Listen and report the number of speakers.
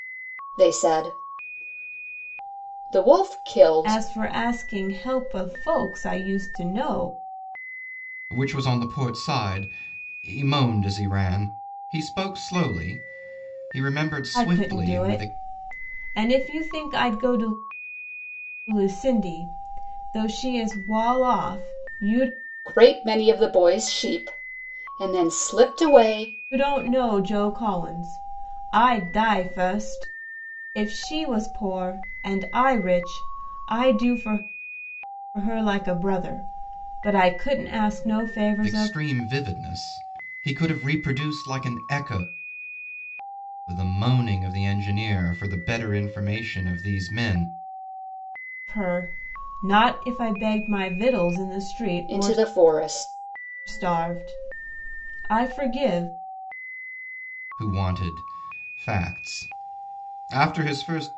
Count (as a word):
three